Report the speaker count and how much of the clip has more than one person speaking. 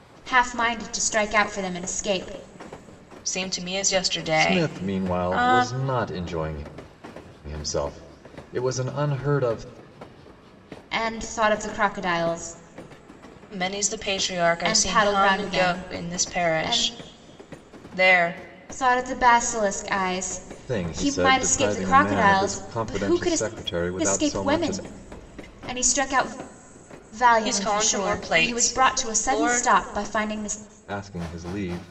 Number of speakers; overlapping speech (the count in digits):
3, about 30%